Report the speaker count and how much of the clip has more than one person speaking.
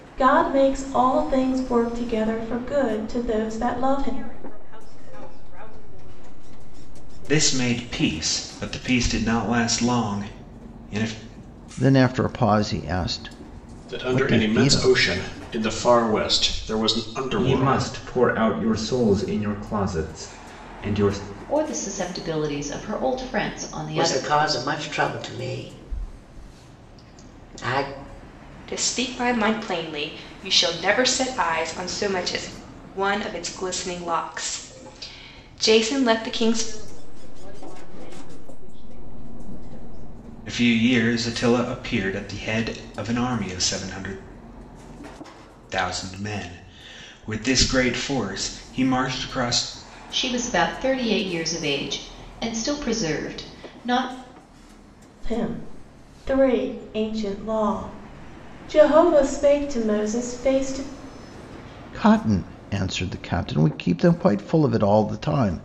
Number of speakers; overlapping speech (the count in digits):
9, about 5%